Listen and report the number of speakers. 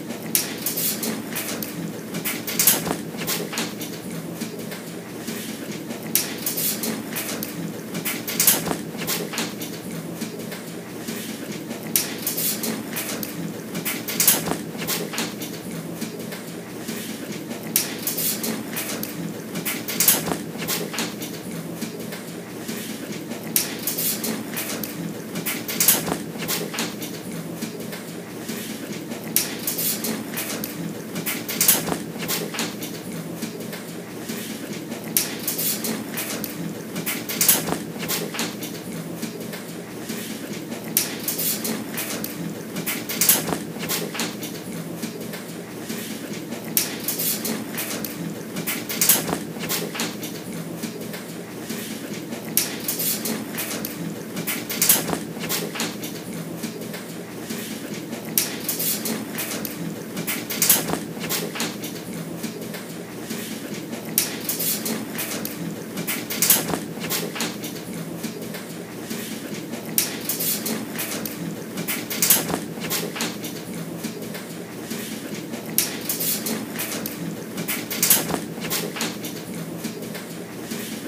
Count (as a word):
zero